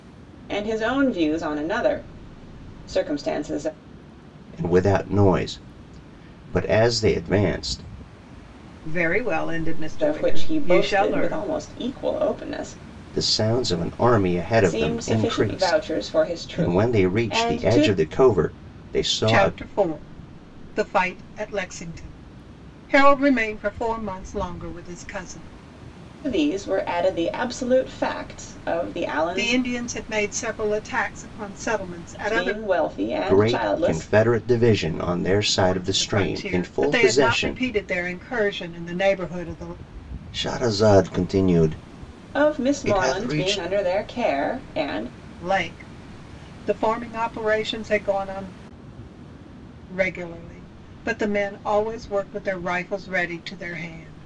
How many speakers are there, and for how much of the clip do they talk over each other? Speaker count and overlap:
3, about 18%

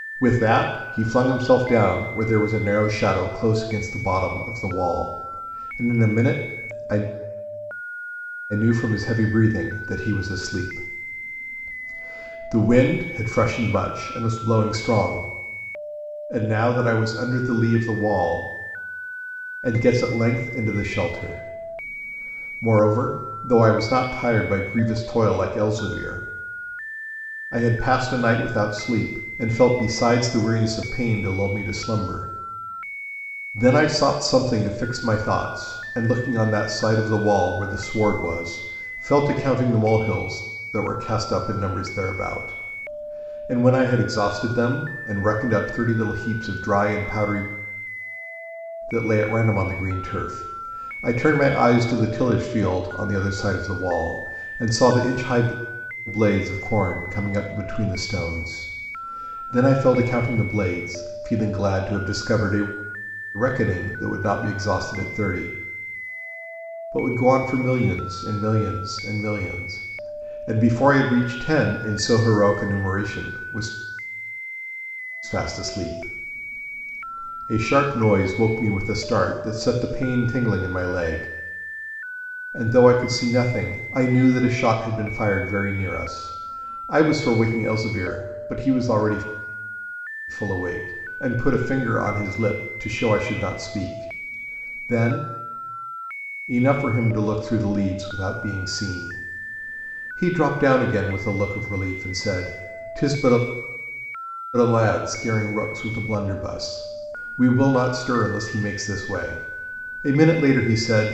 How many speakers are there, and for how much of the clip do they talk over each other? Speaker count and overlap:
1, no overlap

